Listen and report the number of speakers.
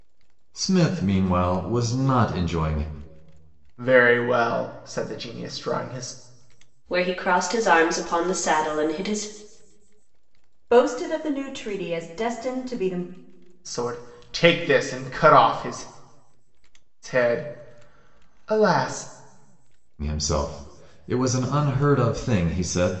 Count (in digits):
4